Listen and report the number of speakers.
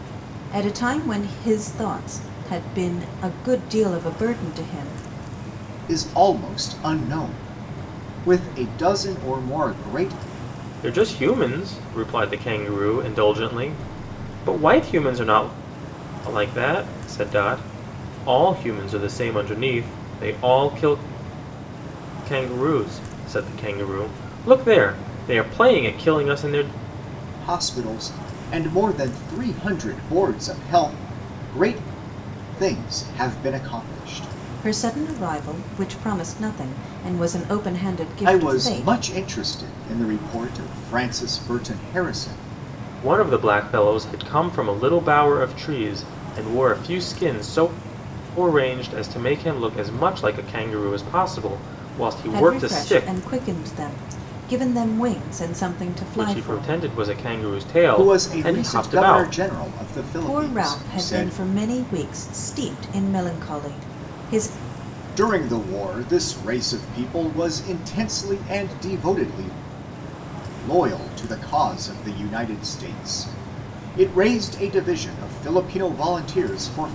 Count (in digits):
3